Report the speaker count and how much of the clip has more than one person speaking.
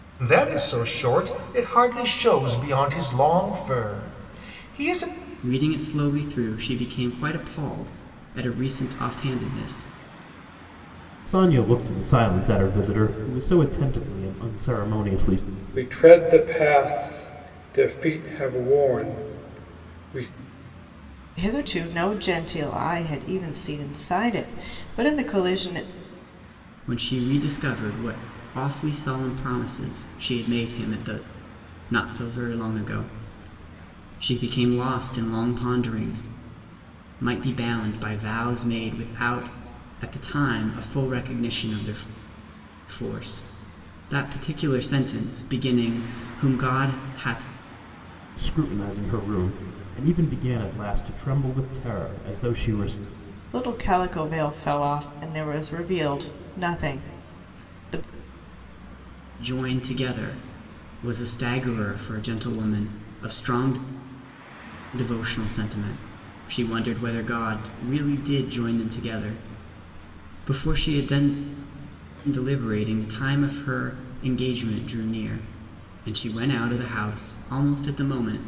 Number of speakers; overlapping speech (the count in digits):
5, no overlap